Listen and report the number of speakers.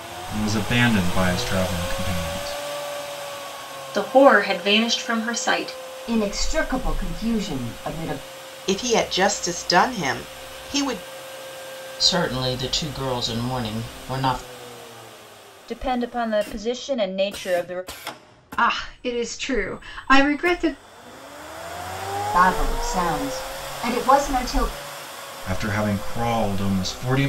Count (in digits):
7